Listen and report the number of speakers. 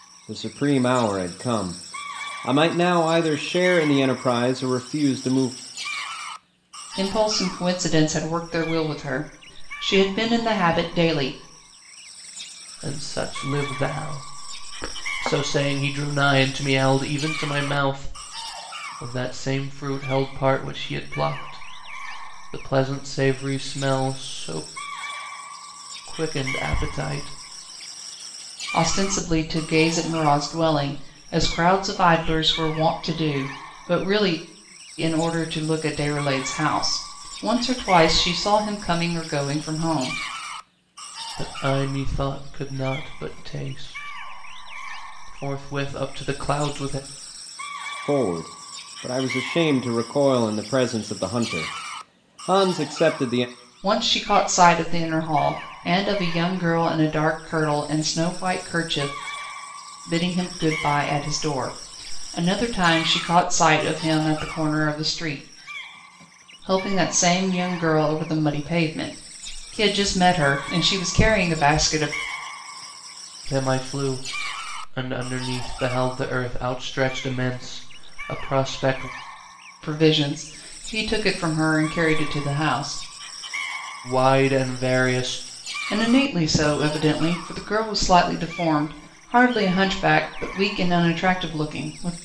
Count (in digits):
3